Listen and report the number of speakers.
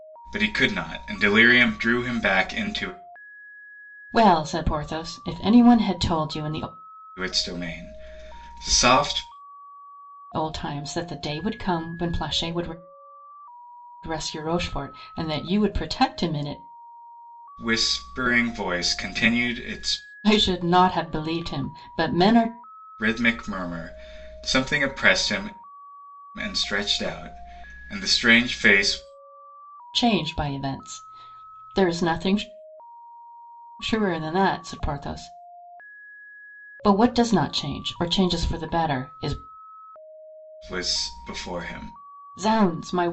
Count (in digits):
2